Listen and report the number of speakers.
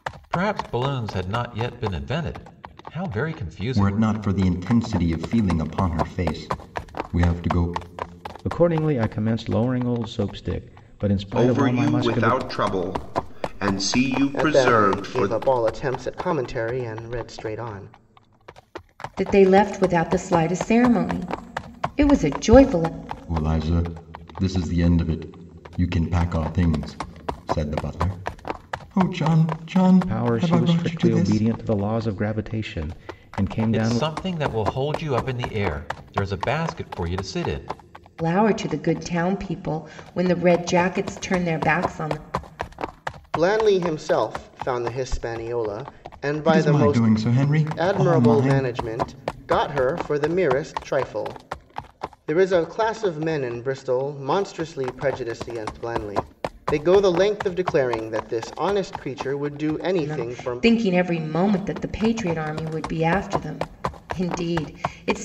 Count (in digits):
6